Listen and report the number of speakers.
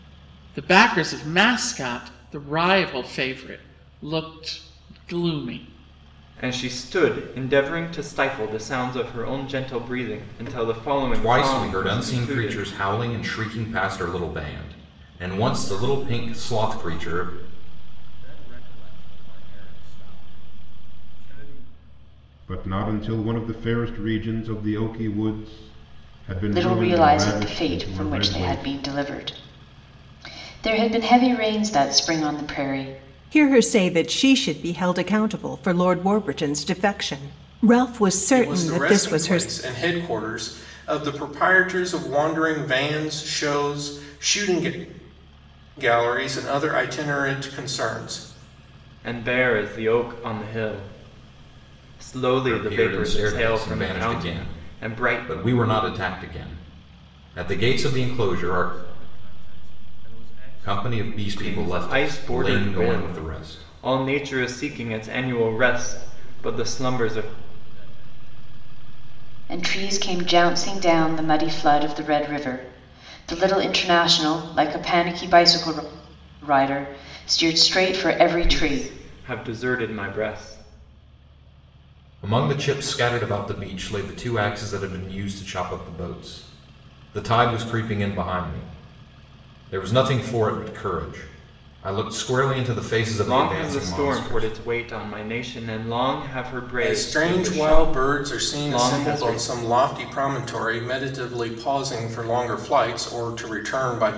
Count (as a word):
eight